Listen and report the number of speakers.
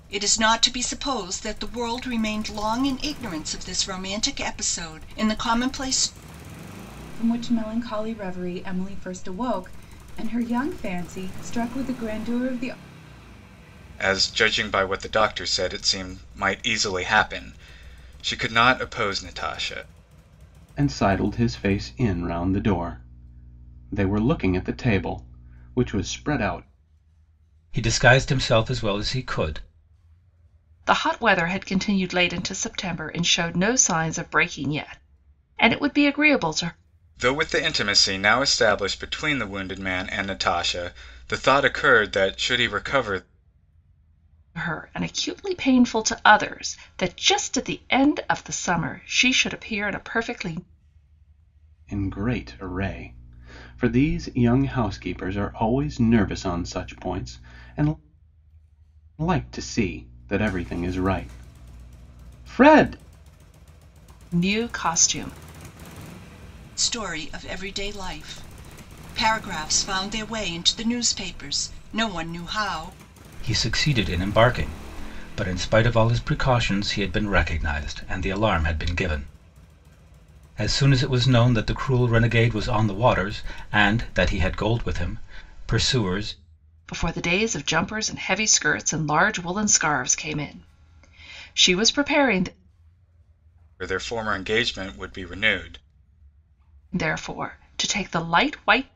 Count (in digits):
6